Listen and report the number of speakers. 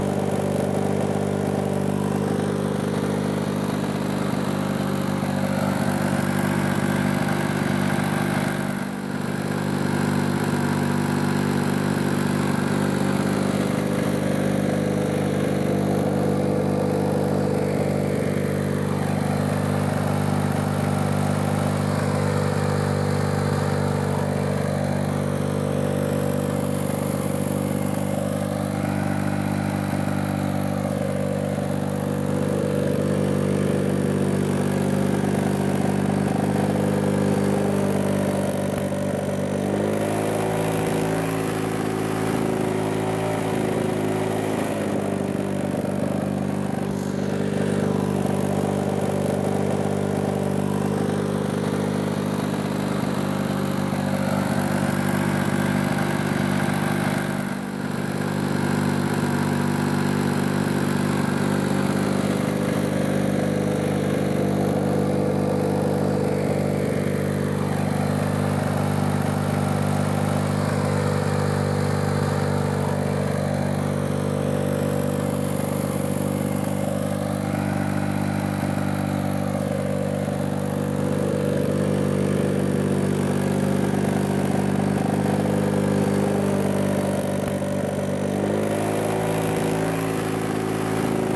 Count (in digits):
0